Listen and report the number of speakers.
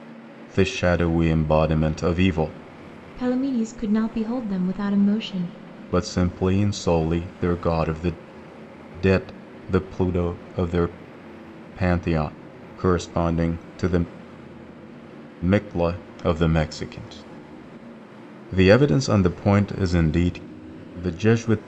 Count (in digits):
2